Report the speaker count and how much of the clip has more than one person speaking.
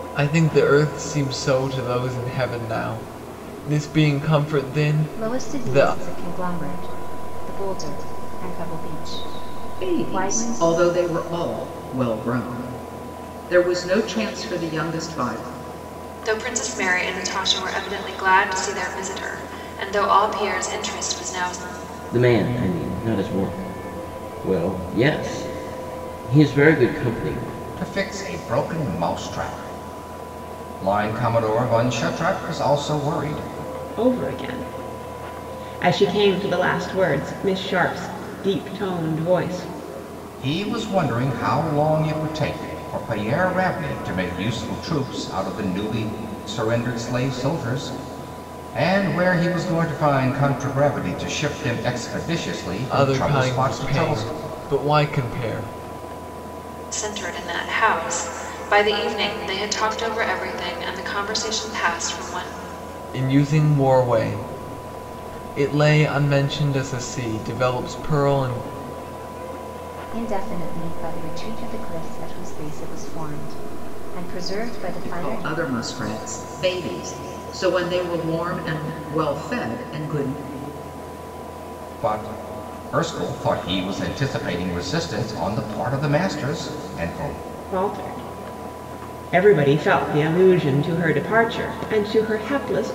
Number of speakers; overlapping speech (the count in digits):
7, about 4%